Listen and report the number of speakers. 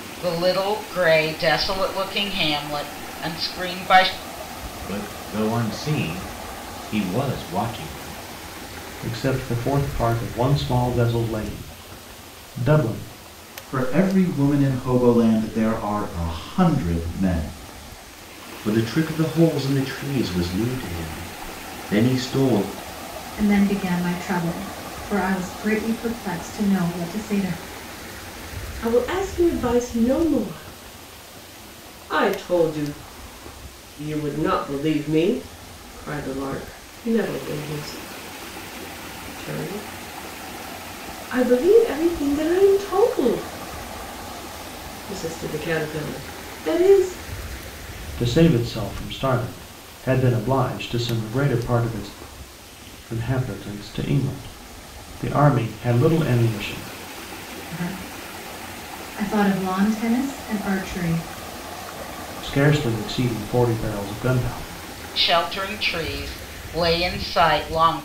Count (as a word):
seven